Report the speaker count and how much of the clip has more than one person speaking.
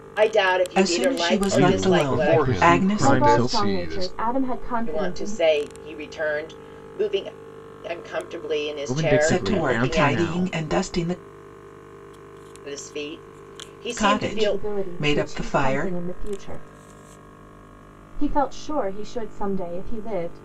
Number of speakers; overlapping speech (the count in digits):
5, about 37%